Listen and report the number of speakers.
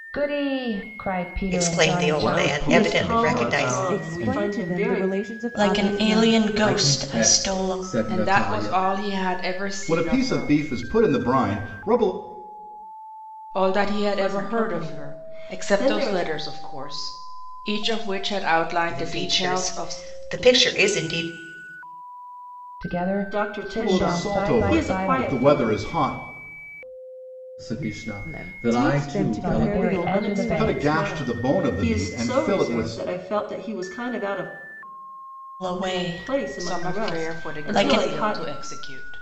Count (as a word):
nine